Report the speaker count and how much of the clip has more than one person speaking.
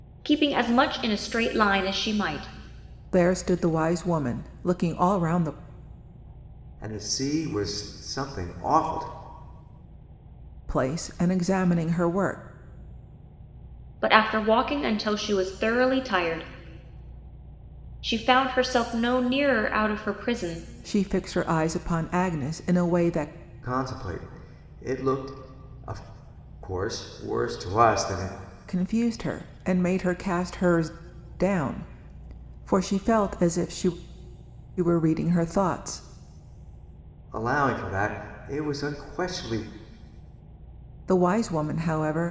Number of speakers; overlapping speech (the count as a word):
three, no overlap